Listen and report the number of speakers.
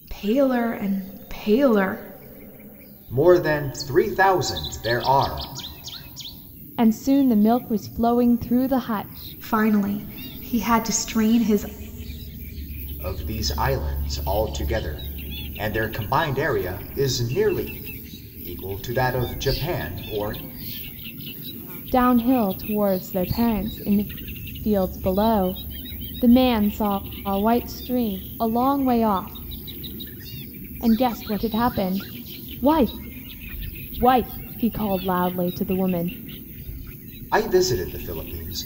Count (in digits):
3